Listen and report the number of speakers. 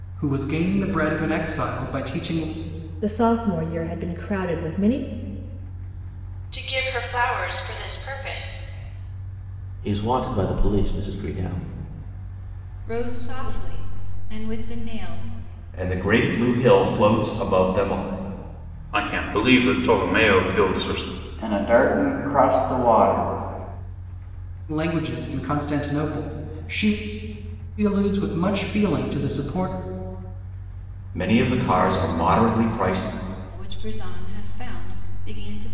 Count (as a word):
eight